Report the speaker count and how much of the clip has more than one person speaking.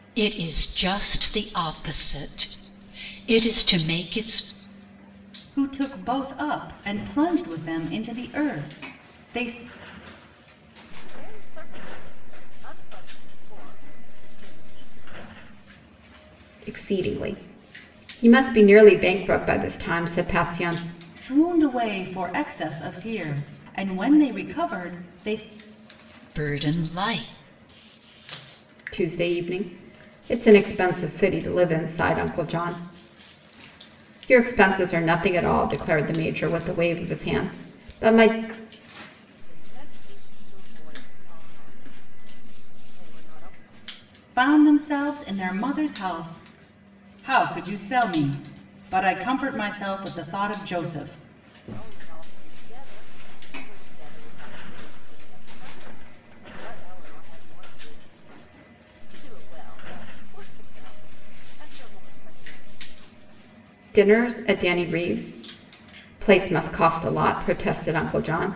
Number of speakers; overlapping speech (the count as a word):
four, no overlap